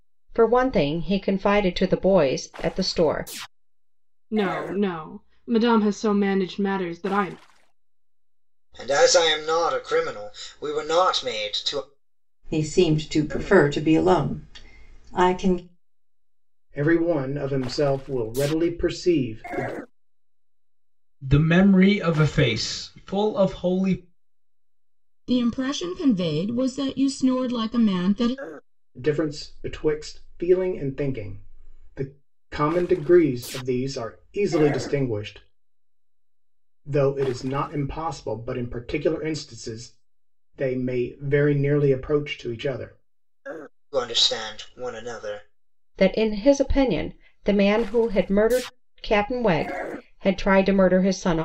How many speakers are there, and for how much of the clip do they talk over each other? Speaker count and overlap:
7, no overlap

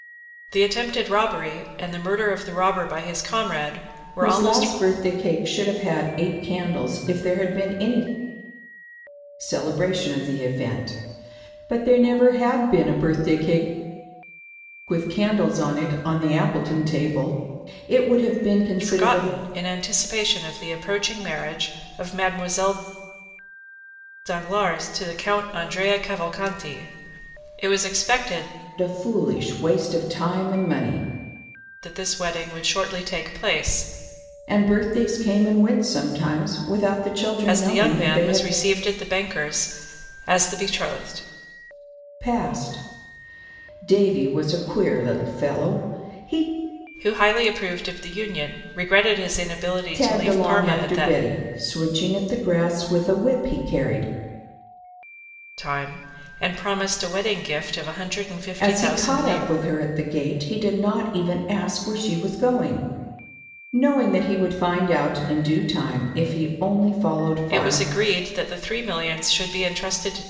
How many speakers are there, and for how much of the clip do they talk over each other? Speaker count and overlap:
2, about 7%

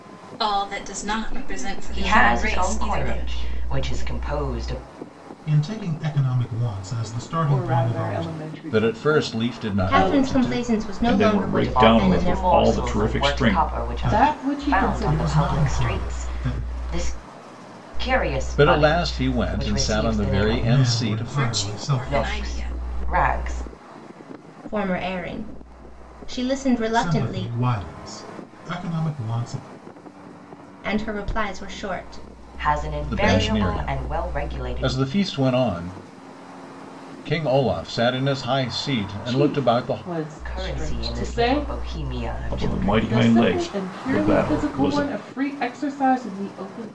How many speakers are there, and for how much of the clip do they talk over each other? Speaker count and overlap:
8, about 50%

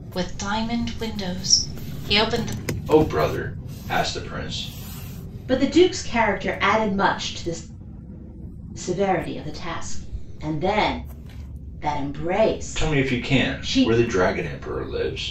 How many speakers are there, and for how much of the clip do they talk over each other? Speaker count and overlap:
3, about 8%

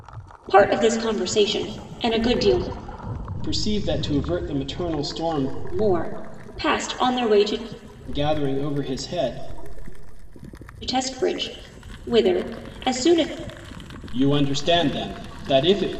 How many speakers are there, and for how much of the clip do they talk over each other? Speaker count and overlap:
2, no overlap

